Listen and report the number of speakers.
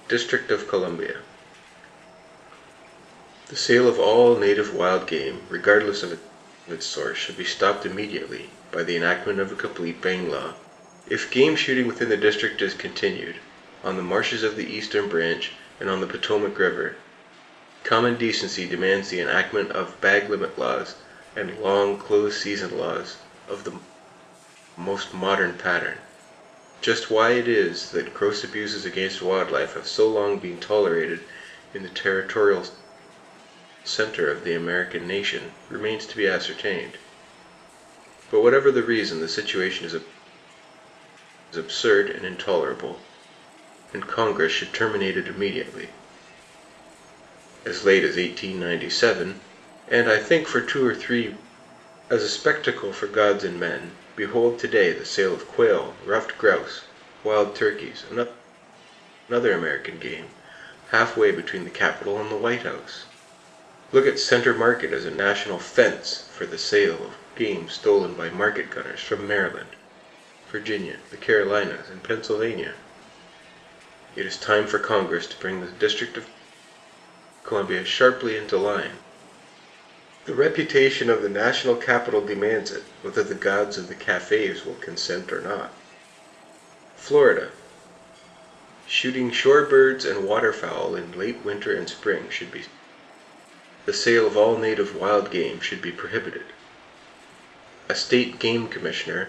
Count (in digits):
1